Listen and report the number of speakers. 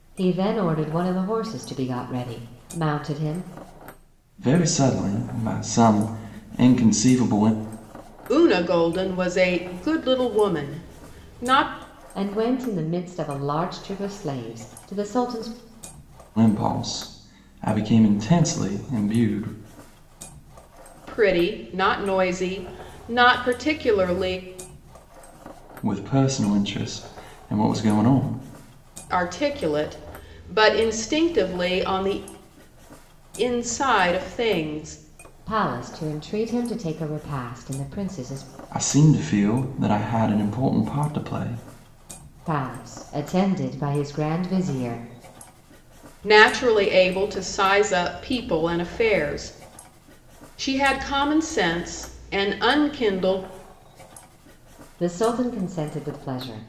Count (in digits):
3